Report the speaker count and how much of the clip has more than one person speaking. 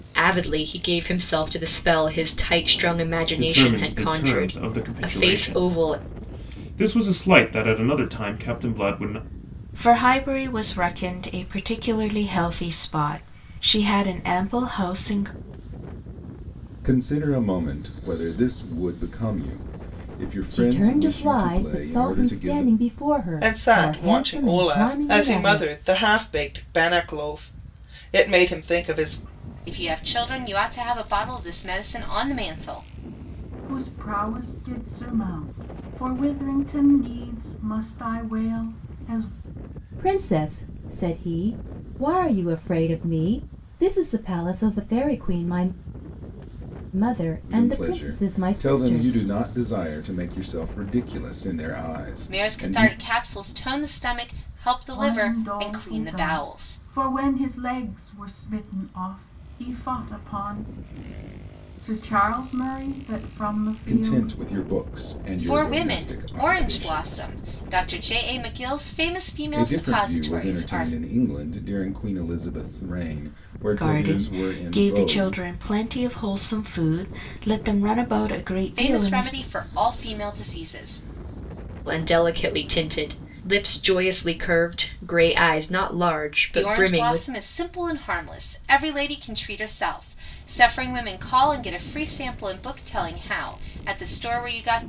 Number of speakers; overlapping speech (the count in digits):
8, about 20%